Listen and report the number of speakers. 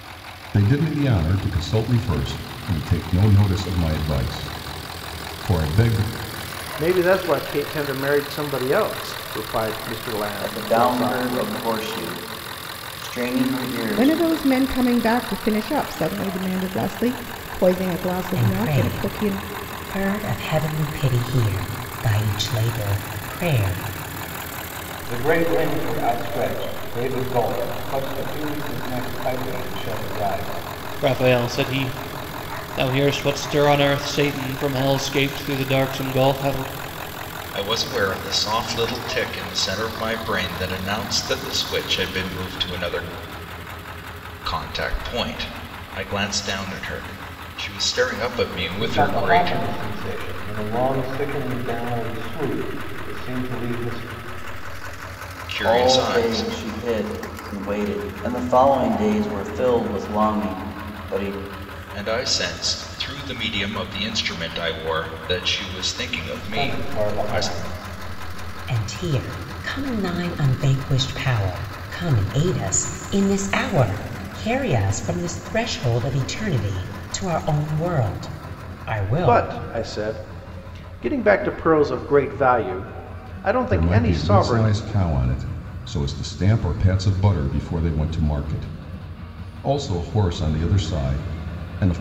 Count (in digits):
8